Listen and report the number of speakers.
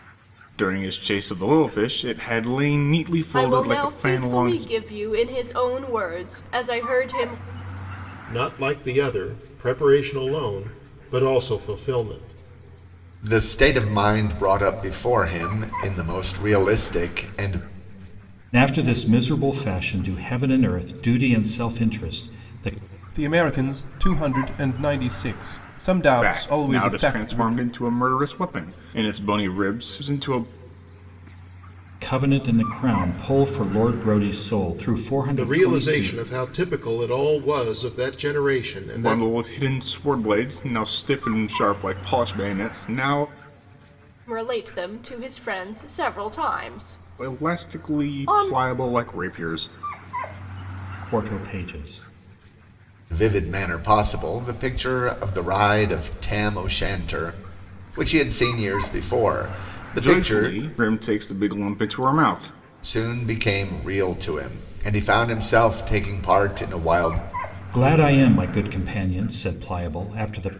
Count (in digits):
6